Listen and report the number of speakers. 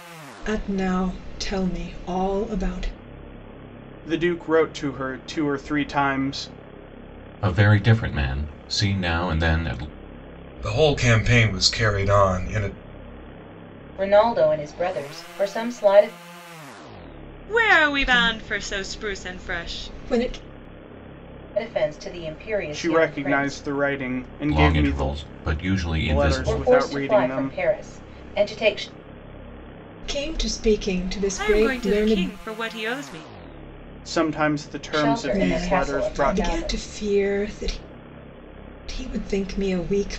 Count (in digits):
6